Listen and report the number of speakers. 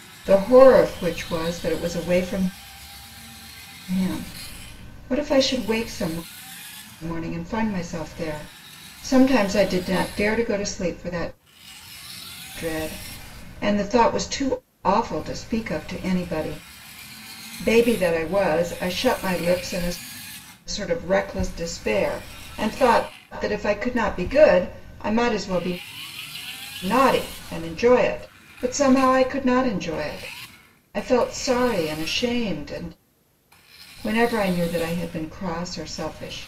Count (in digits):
1